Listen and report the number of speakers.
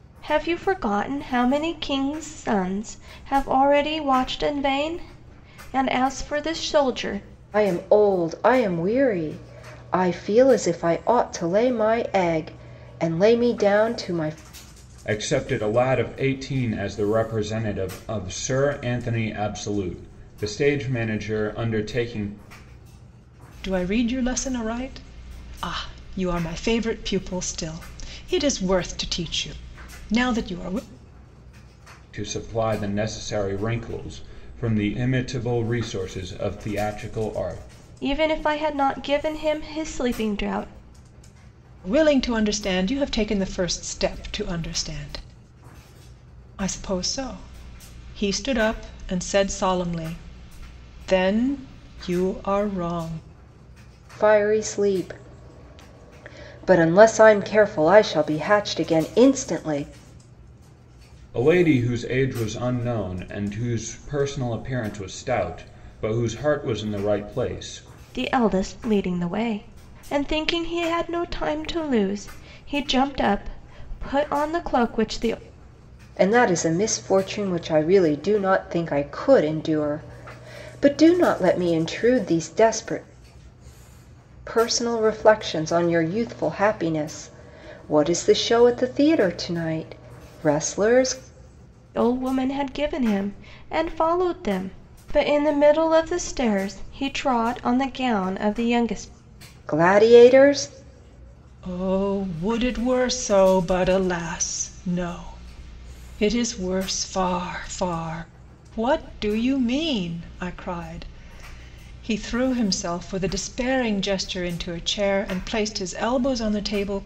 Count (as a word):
four